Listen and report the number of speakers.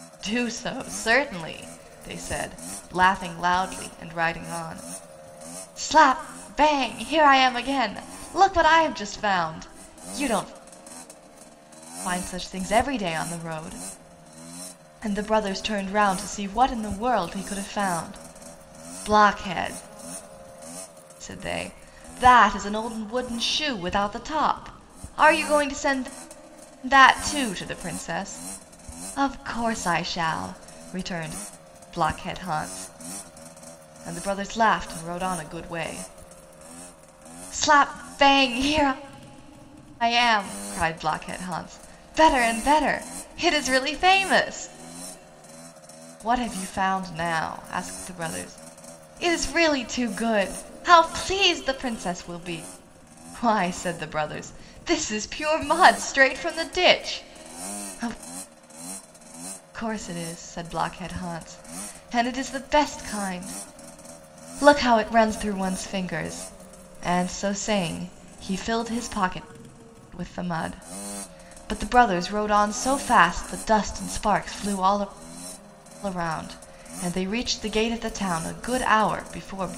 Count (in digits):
1